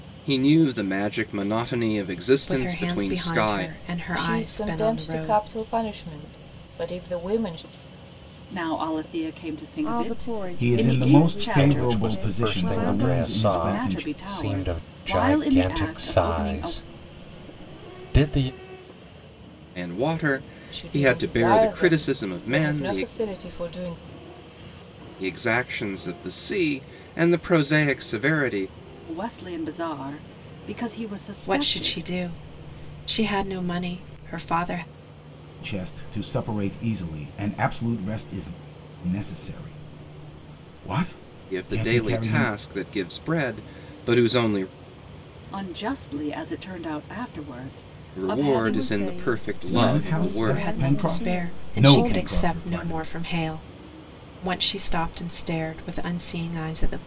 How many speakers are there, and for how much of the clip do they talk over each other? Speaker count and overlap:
7, about 32%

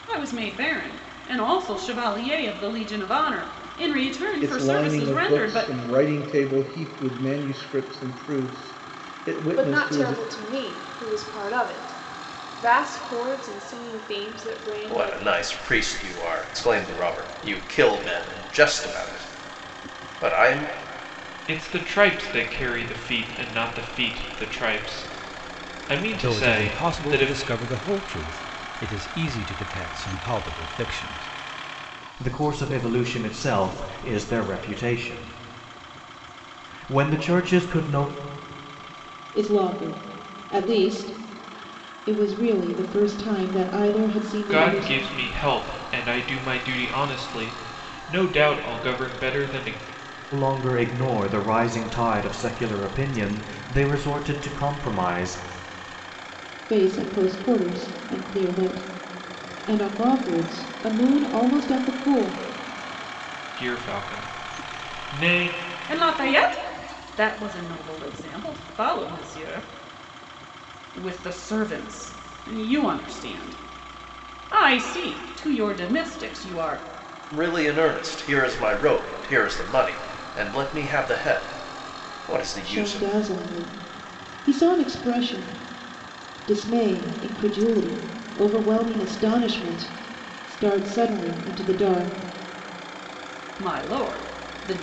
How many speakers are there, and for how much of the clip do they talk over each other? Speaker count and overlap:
8, about 5%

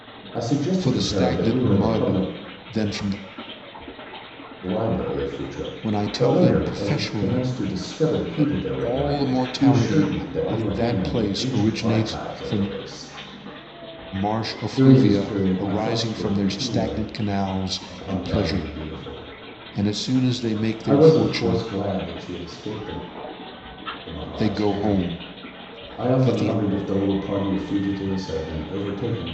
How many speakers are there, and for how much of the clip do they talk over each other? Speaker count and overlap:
2, about 45%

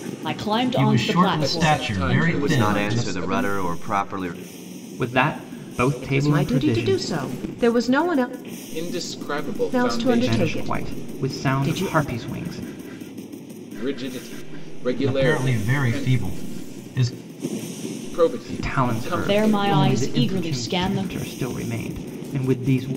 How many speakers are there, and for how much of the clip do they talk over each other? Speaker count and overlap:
6, about 43%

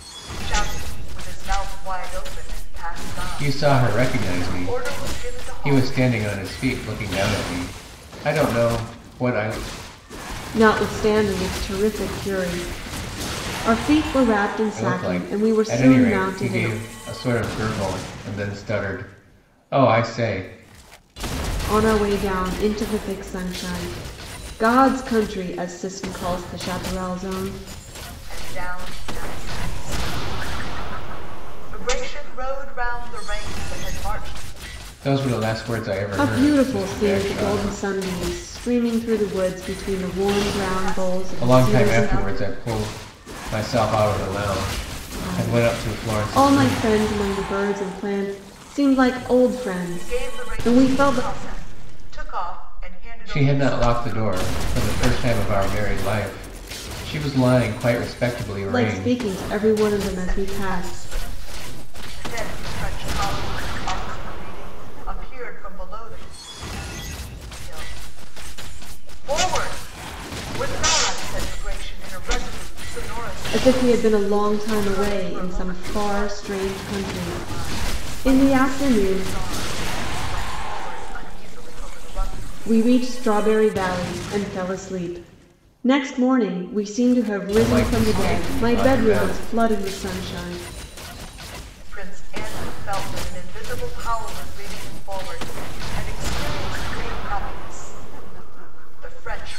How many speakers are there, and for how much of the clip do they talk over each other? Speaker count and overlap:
3, about 24%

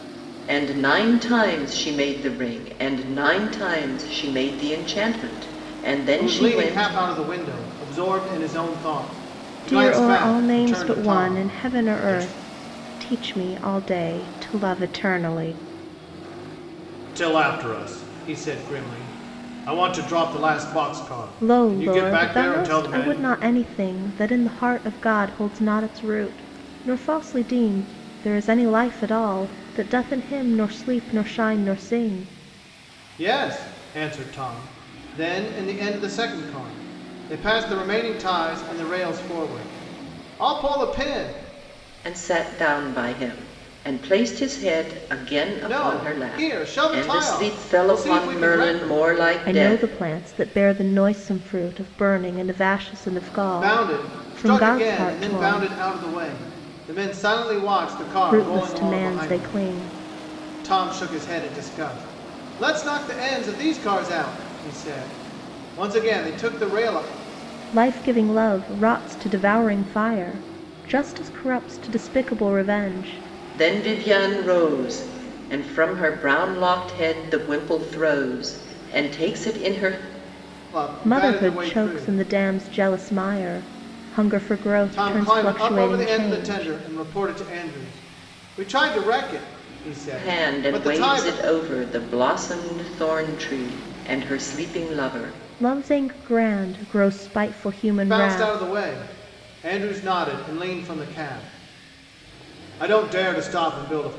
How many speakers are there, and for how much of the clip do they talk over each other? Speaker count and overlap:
3, about 17%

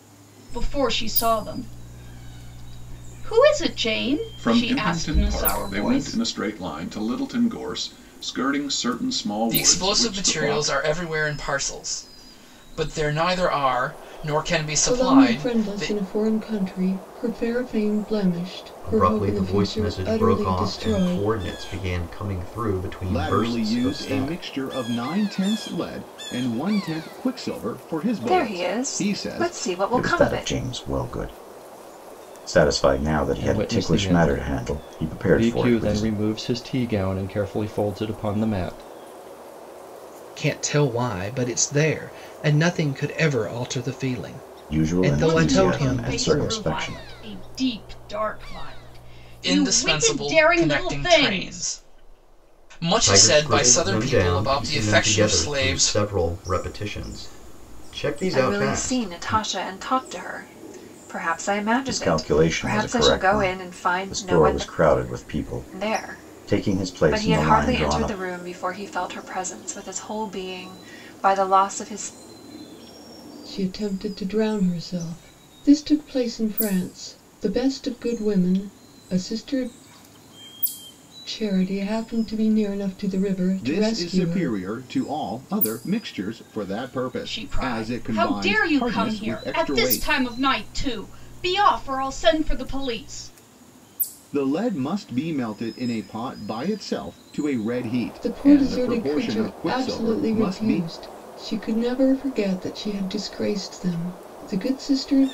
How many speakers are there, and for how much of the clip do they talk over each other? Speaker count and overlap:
10, about 32%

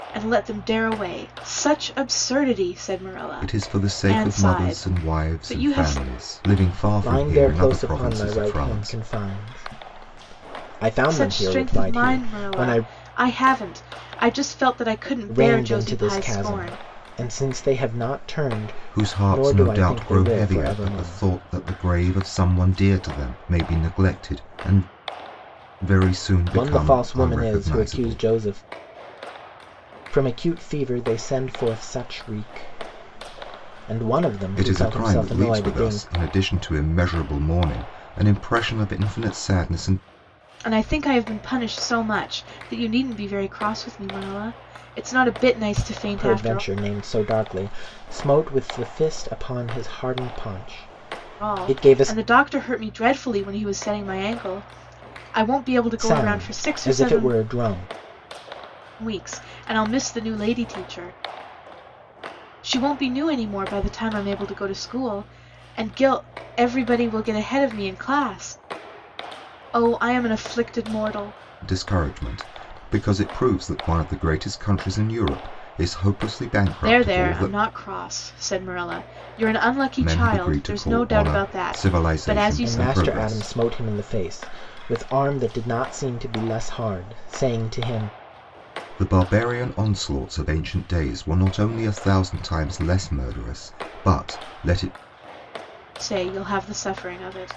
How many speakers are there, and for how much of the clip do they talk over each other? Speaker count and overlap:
3, about 21%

